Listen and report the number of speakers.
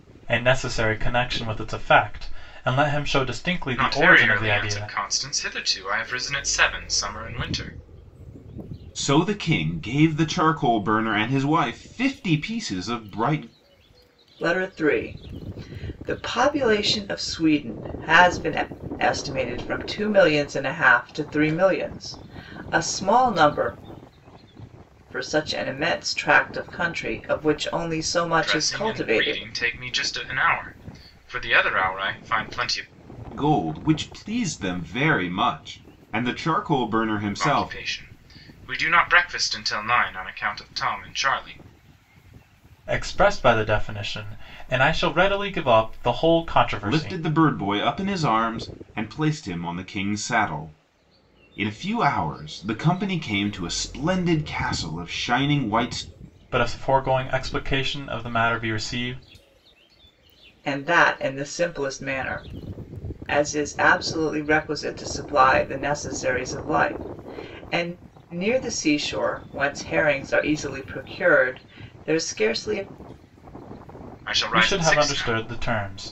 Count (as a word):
four